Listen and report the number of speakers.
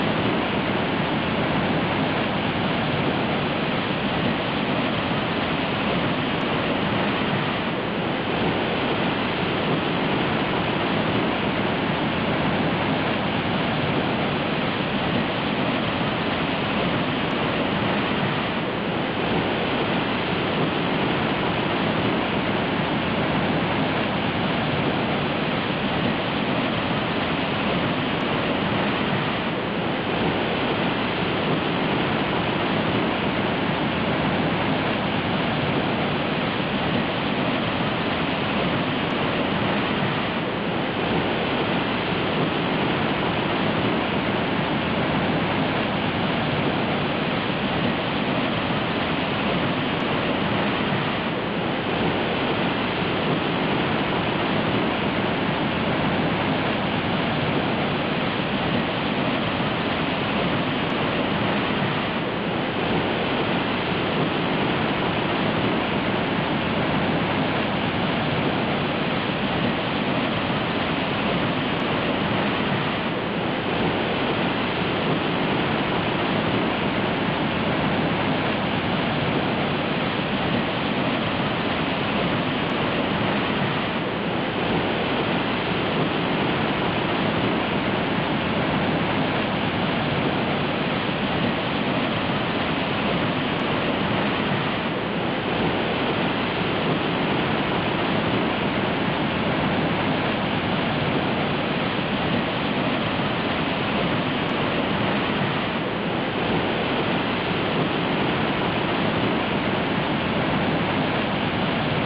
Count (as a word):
zero